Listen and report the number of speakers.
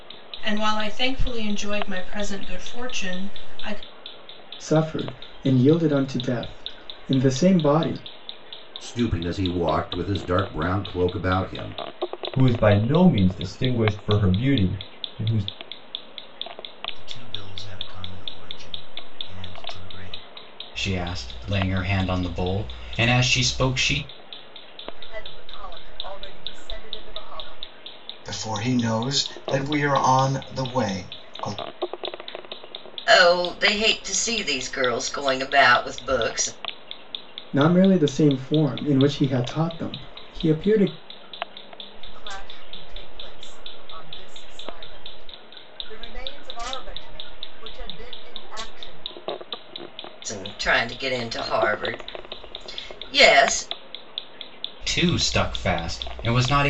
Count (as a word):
nine